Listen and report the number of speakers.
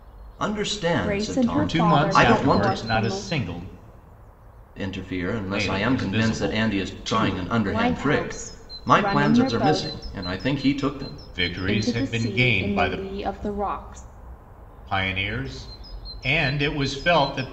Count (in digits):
3